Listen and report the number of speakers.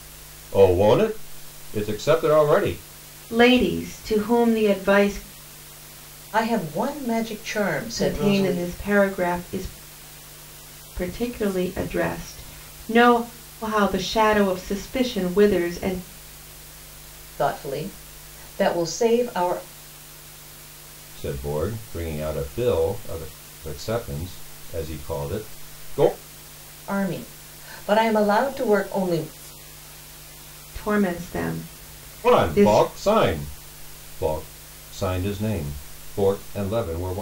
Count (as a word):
three